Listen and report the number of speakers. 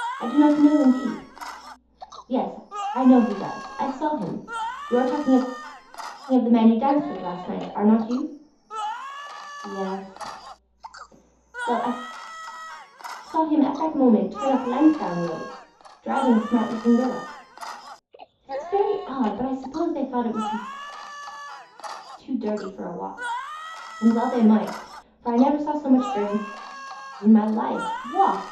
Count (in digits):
1